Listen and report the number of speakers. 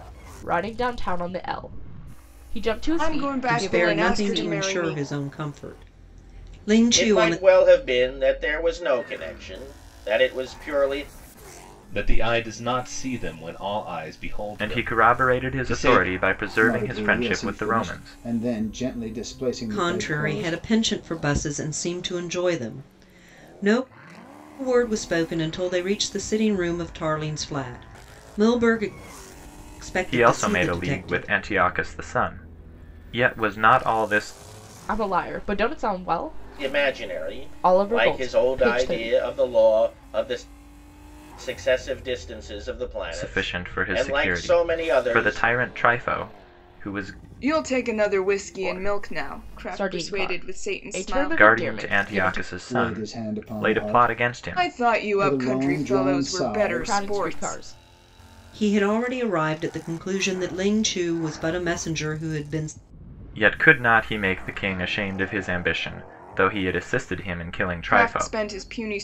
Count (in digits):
7